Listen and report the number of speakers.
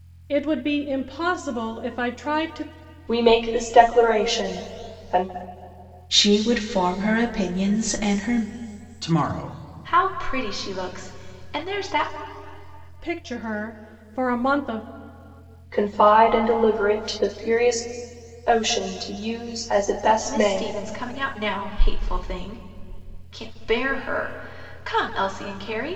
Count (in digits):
5